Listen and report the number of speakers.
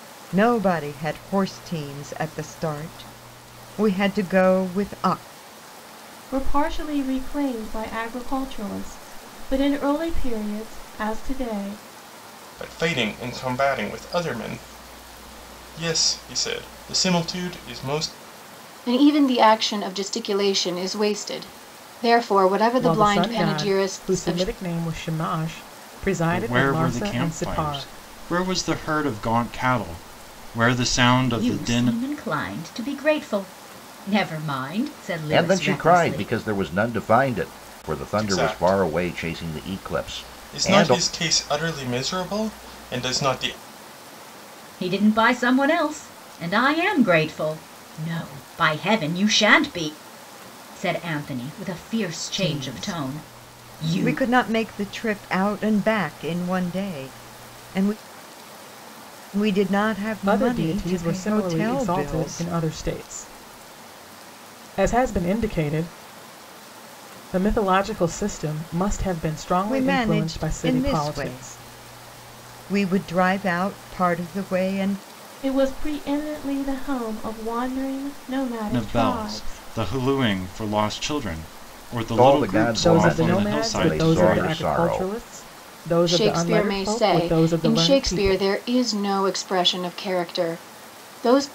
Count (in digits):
8